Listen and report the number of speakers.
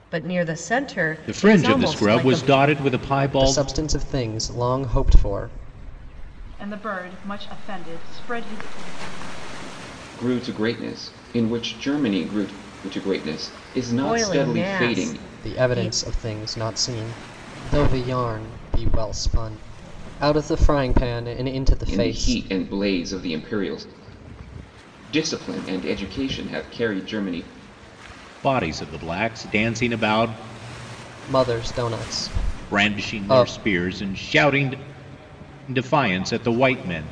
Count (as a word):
five